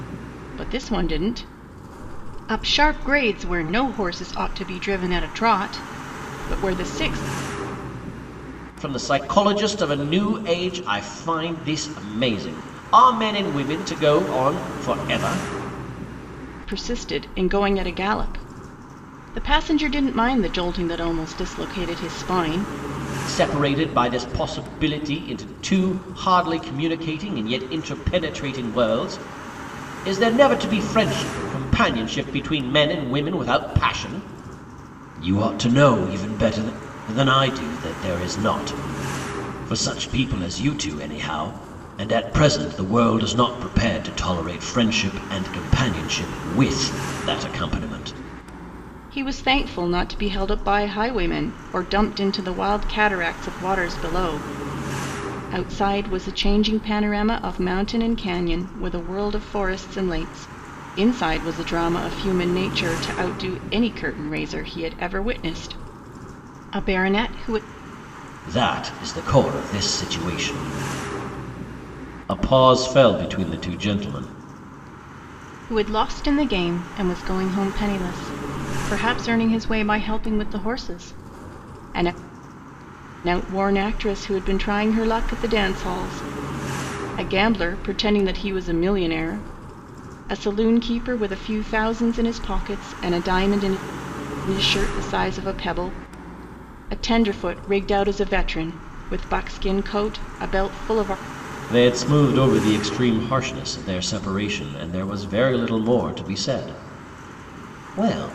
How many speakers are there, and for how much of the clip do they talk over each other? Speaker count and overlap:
2, no overlap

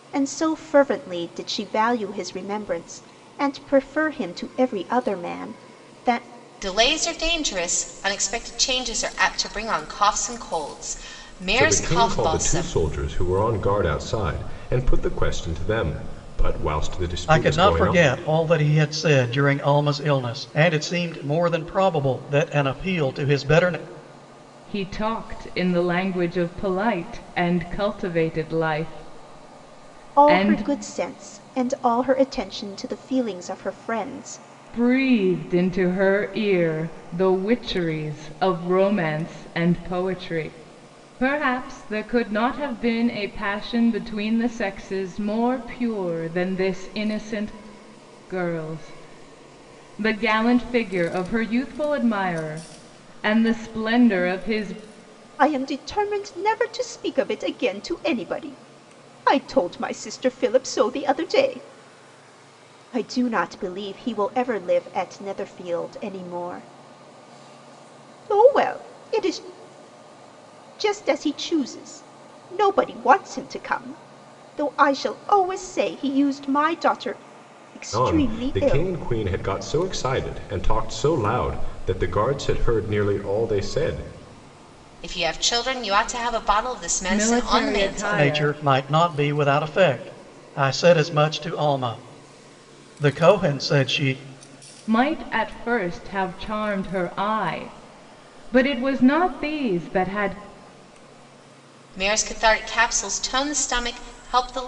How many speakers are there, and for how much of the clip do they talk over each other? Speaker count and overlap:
5, about 5%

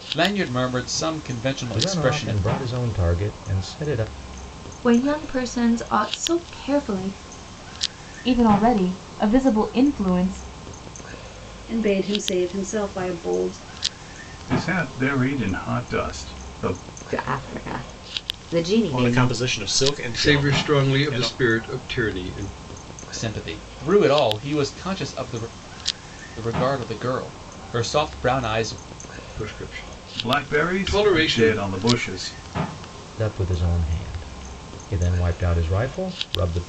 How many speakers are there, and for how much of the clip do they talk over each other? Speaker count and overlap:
9, about 10%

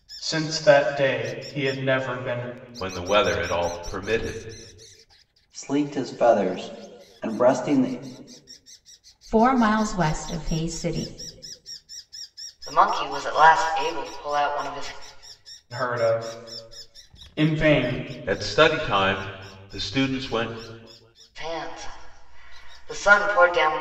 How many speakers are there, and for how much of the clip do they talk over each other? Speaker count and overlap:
5, no overlap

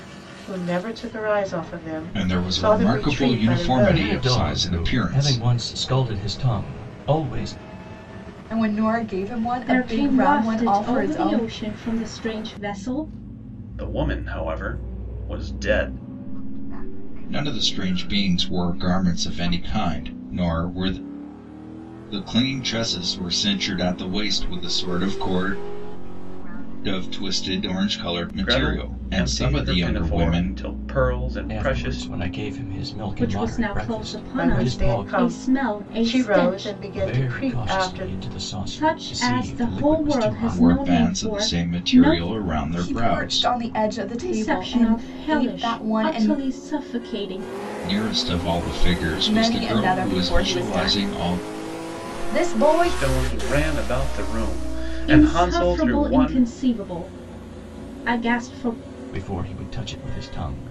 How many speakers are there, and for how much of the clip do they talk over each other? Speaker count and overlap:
7, about 51%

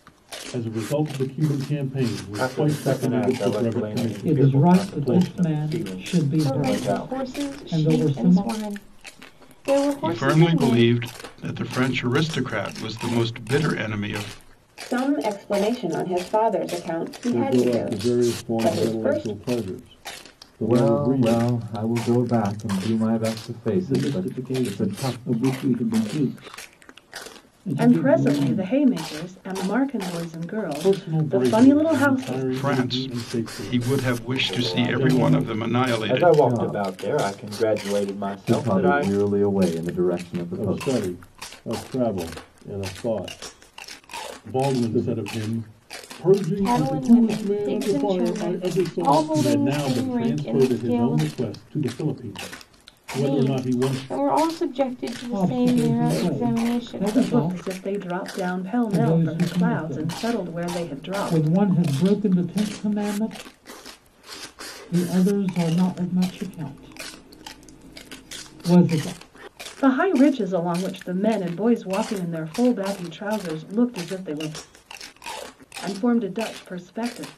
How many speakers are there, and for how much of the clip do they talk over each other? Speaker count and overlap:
10, about 42%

